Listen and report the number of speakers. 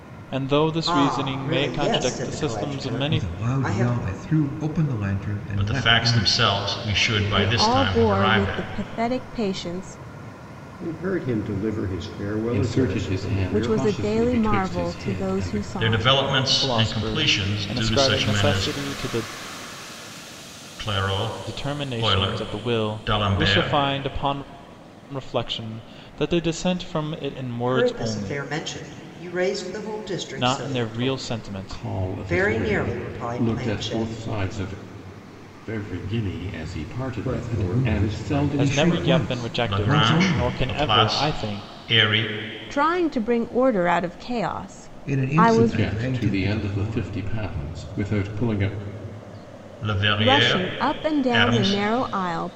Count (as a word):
seven